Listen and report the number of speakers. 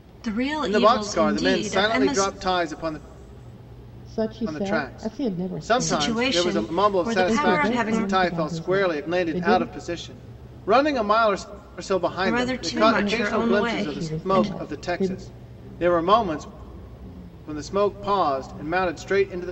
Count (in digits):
3